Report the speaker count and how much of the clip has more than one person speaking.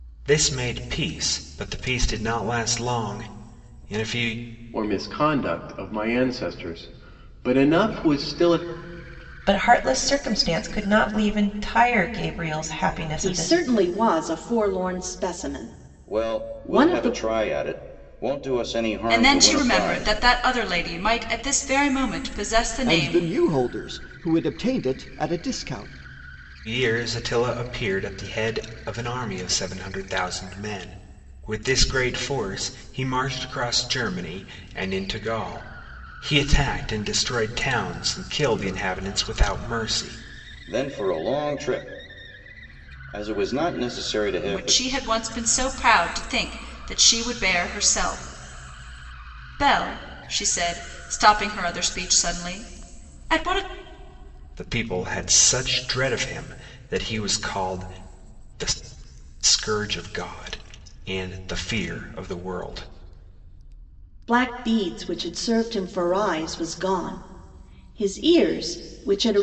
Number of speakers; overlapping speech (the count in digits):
7, about 5%